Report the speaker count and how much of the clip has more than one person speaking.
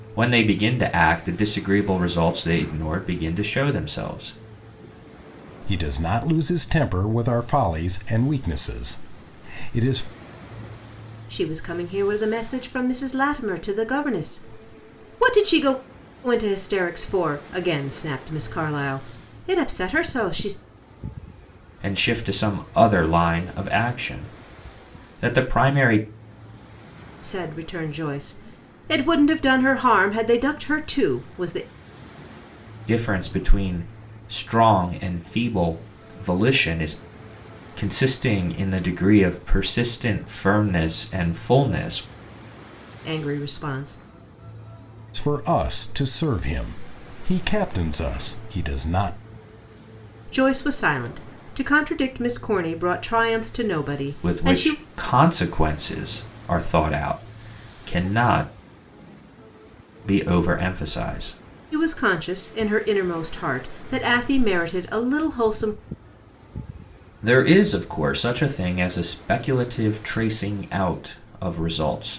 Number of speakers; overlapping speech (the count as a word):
three, about 1%